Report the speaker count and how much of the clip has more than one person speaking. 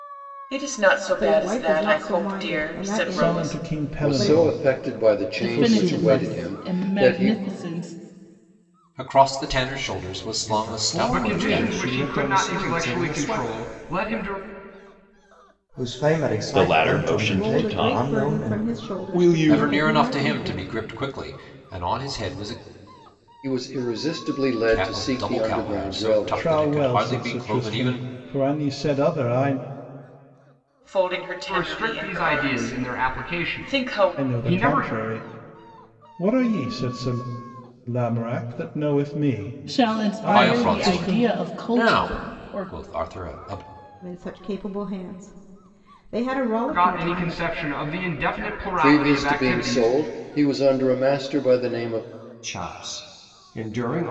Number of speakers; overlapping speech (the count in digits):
10, about 47%